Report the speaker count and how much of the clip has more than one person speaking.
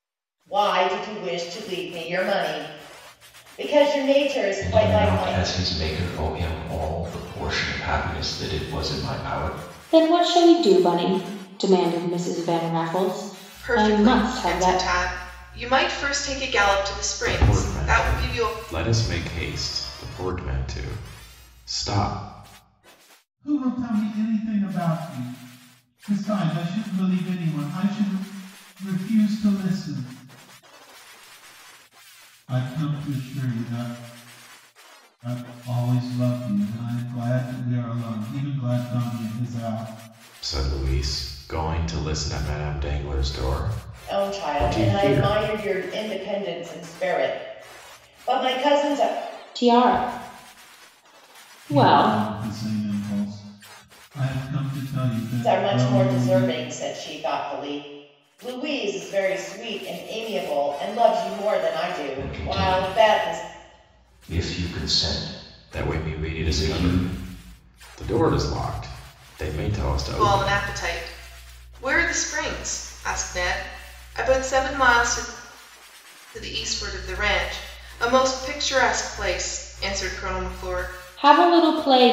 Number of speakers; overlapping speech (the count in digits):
6, about 12%